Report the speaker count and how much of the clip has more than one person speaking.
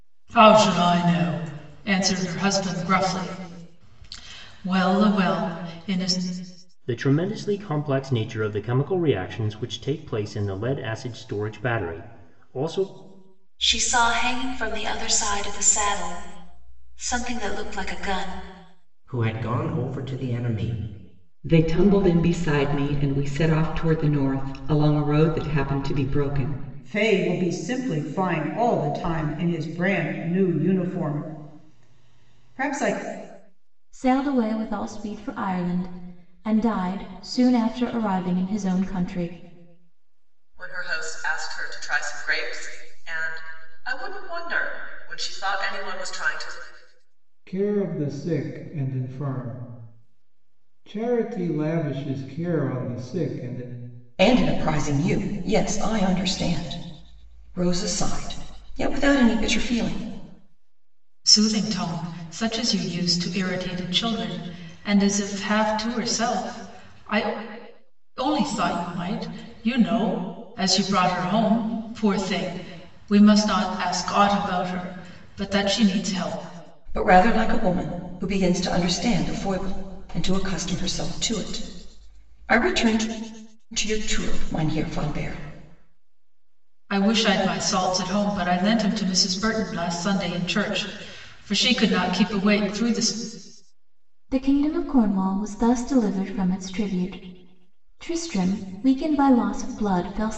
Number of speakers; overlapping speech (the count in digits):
10, no overlap